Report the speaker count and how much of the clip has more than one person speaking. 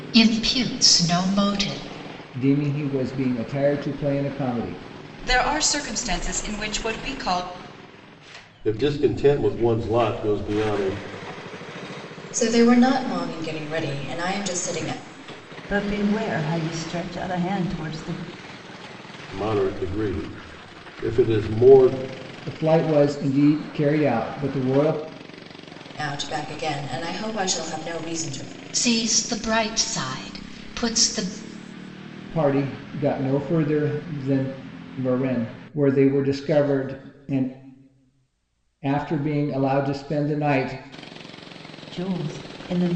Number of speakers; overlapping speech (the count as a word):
six, no overlap